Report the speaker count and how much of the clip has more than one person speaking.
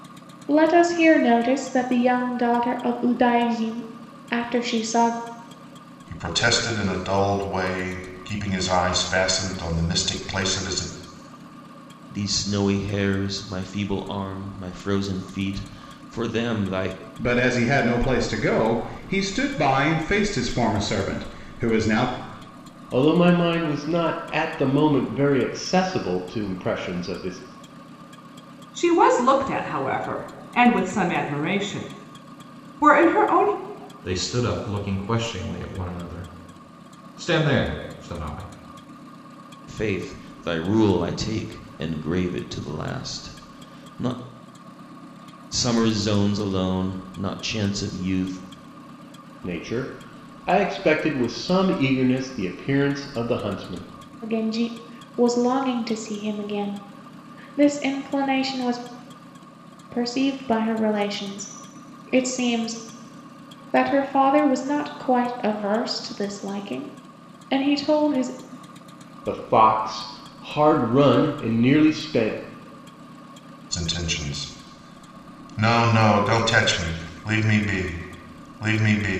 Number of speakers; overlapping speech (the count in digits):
7, no overlap